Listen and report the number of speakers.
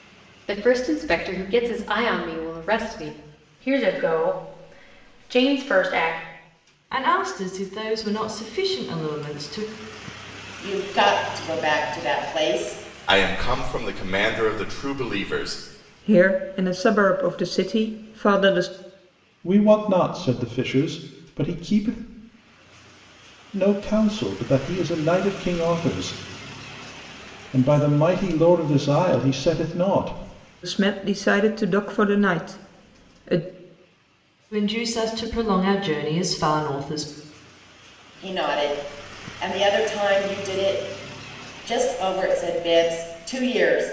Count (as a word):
seven